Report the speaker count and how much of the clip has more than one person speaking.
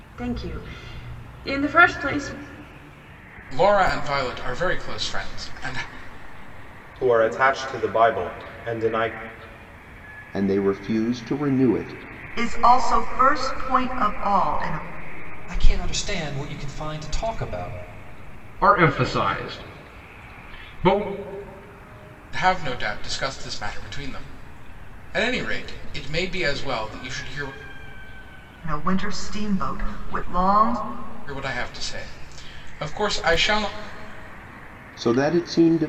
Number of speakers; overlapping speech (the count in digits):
7, no overlap